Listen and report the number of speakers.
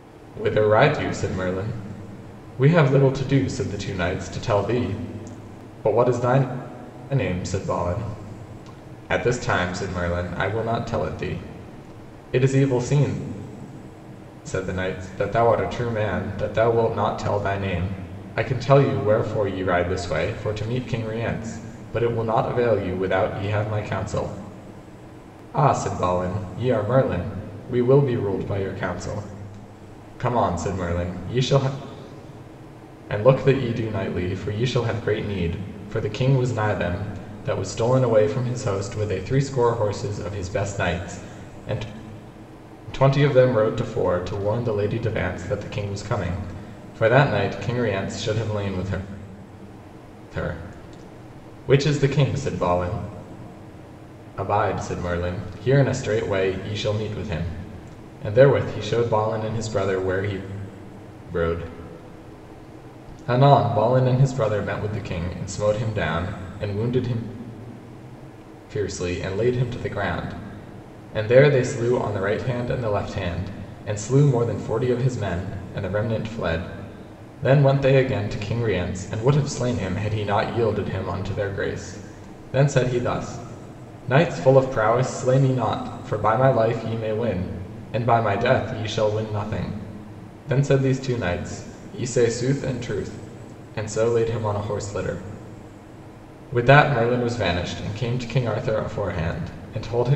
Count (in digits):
1